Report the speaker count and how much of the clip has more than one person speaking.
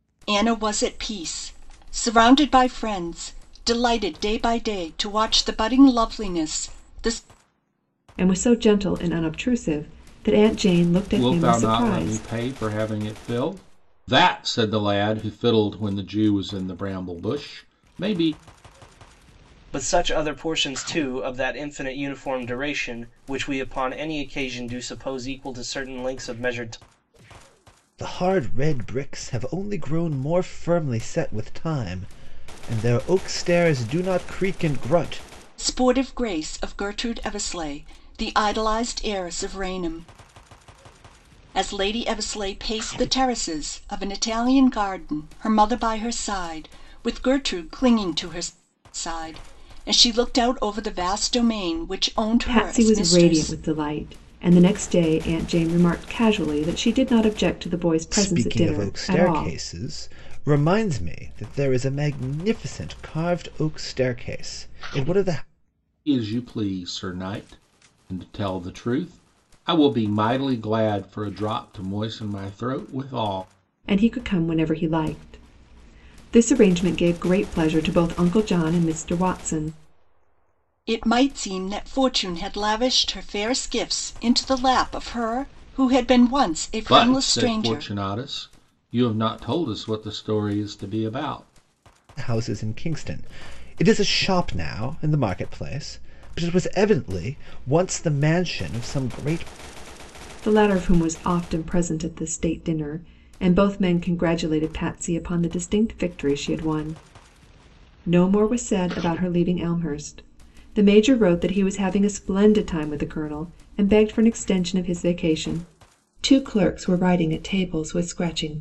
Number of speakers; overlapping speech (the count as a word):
five, about 4%